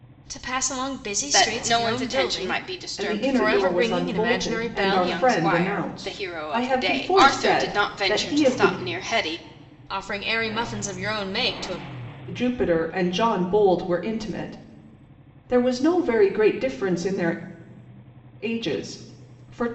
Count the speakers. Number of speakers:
three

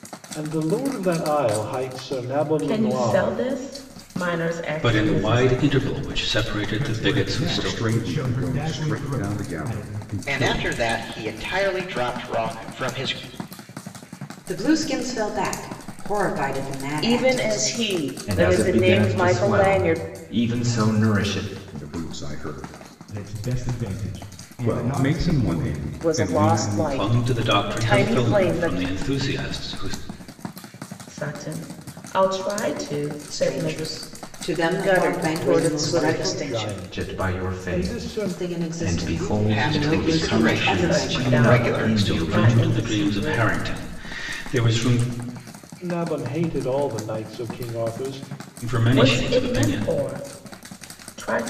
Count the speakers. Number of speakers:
nine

